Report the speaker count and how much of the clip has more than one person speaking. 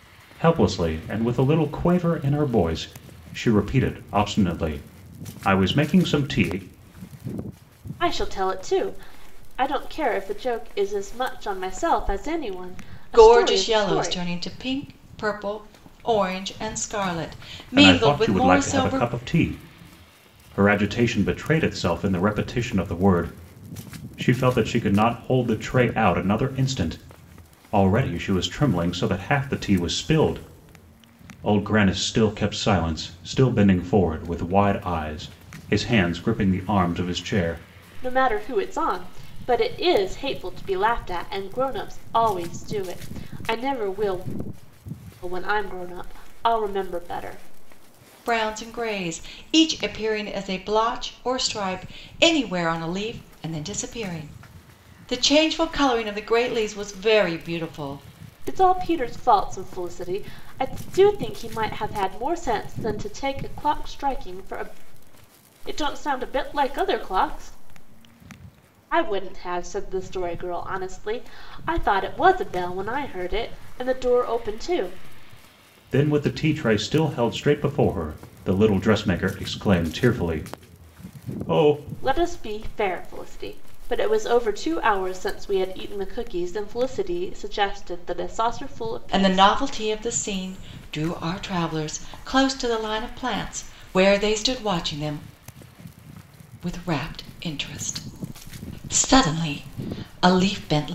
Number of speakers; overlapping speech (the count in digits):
3, about 3%